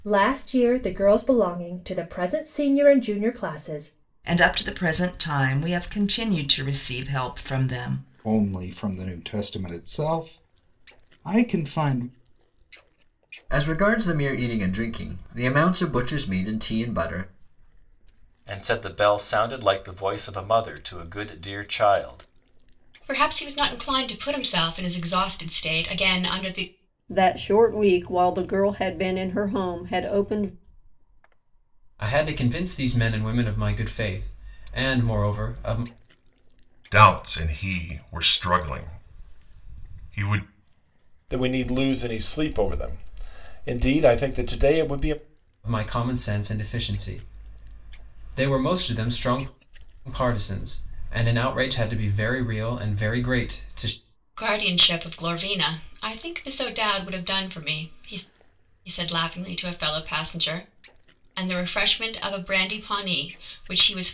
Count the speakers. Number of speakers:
ten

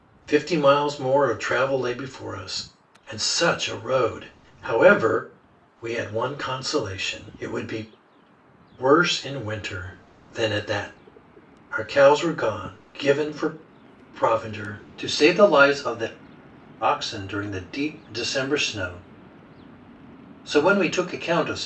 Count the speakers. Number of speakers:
one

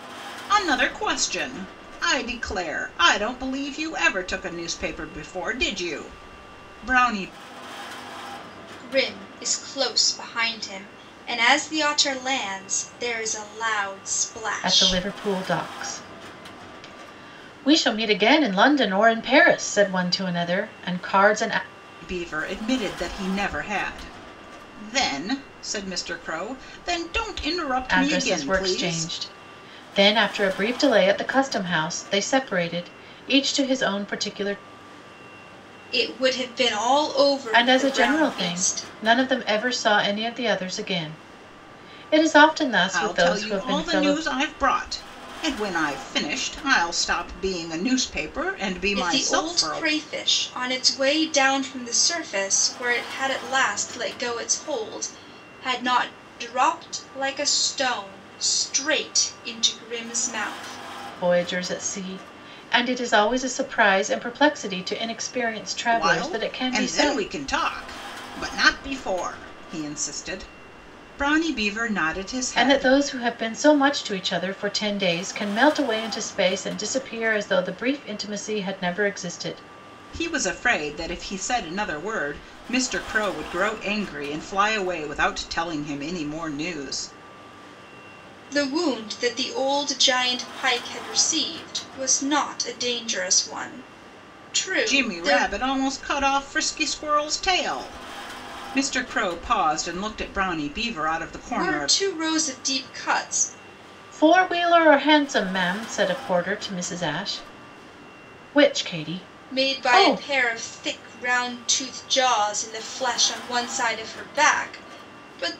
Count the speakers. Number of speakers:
three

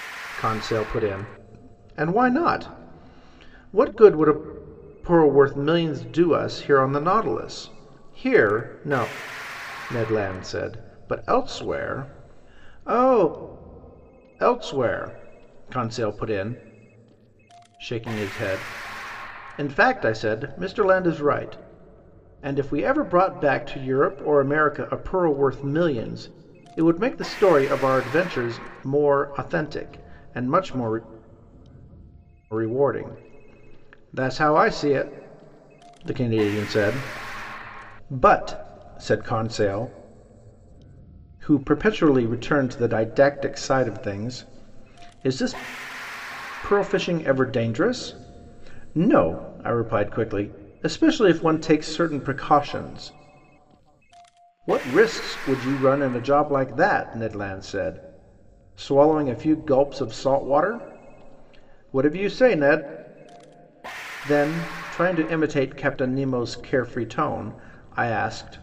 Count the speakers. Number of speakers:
one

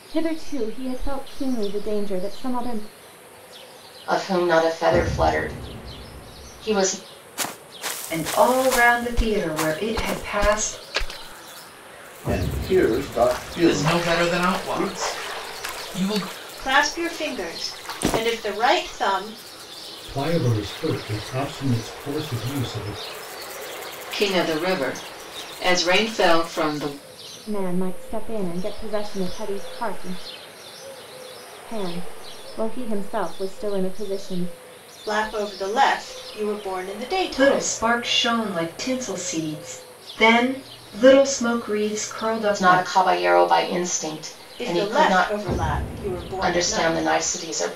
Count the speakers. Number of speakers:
eight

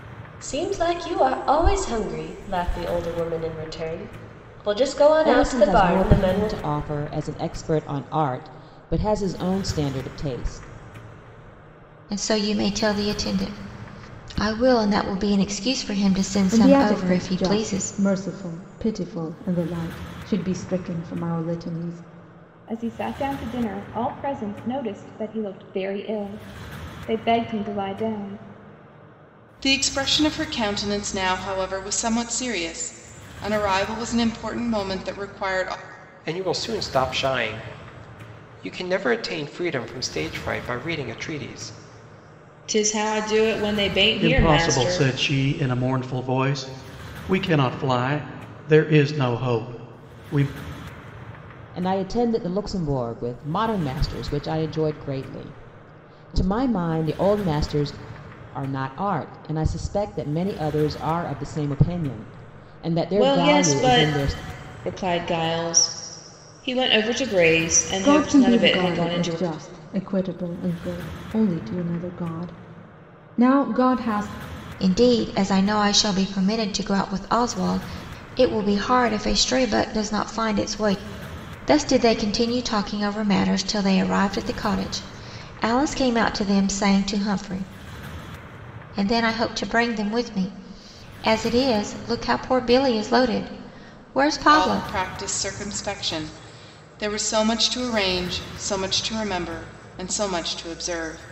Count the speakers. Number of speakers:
nine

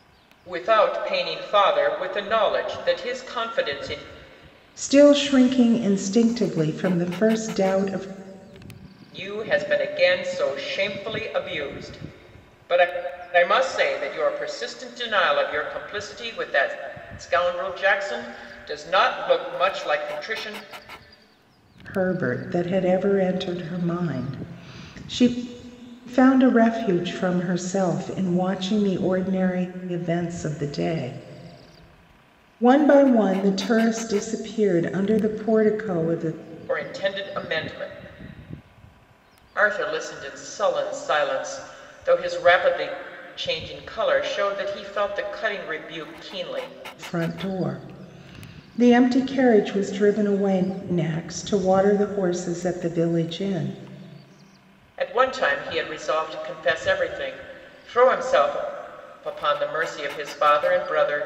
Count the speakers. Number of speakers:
two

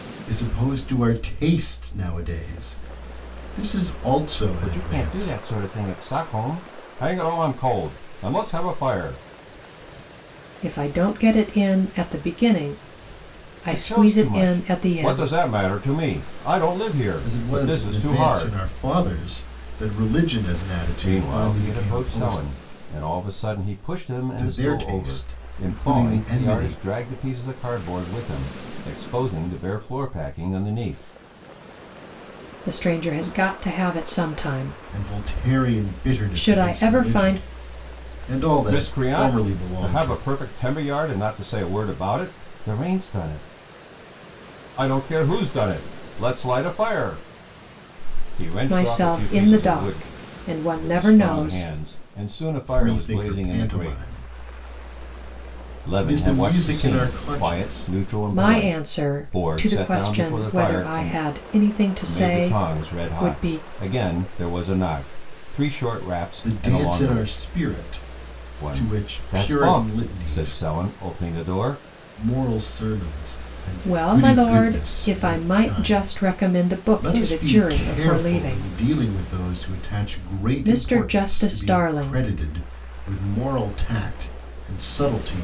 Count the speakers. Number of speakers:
three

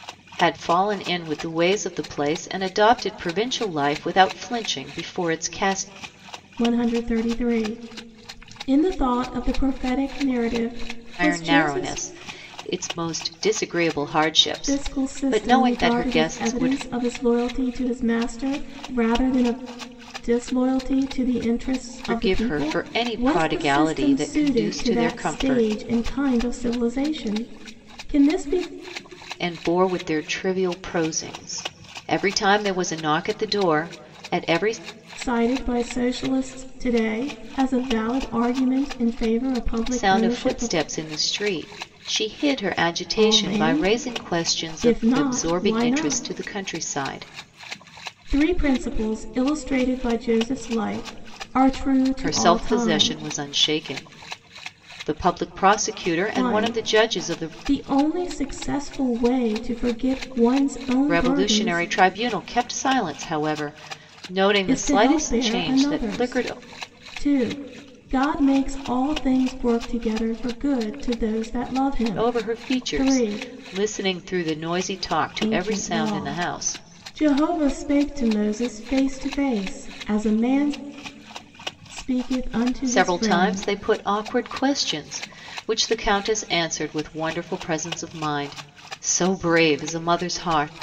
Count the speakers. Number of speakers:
two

